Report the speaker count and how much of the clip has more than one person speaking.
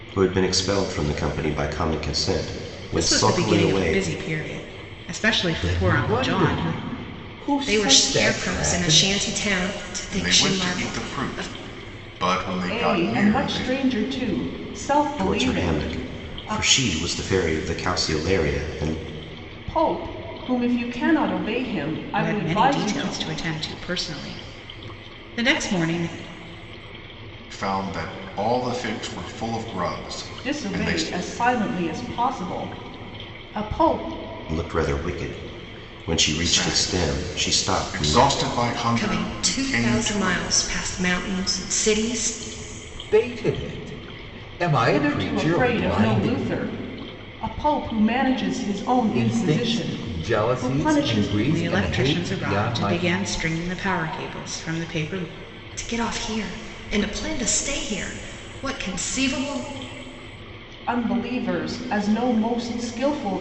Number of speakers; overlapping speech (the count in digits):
6, about 29%